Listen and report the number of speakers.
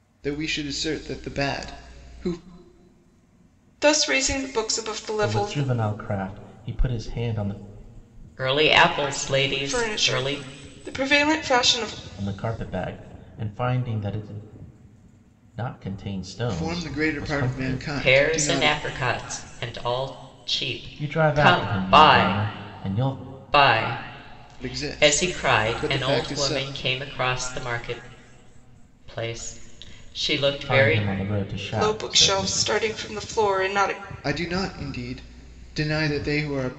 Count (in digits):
4